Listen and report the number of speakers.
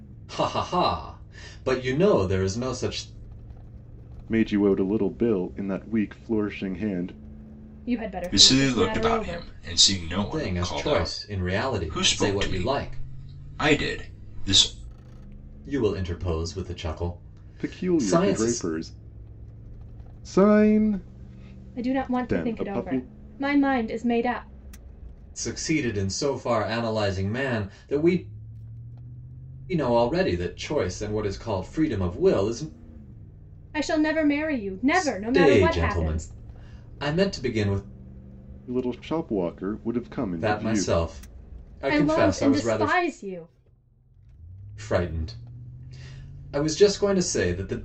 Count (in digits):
4